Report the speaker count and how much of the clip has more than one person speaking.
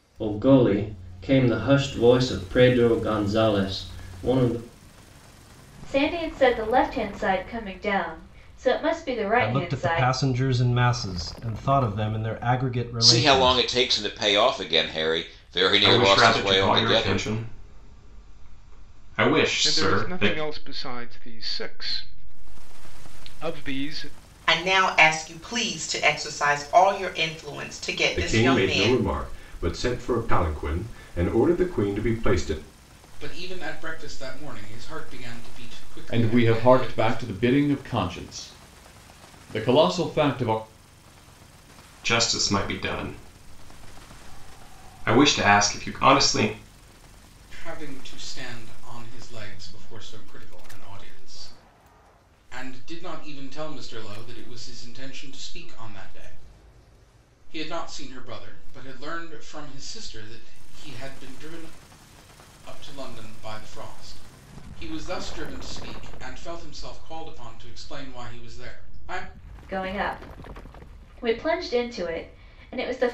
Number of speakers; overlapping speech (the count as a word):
ten, about 8%